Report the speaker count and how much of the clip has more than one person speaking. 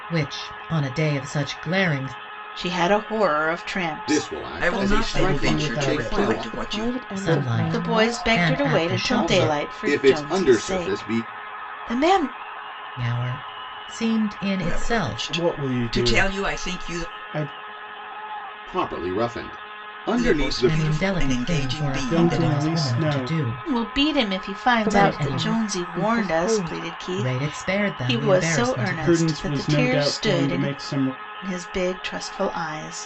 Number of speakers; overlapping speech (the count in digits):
6, about 59%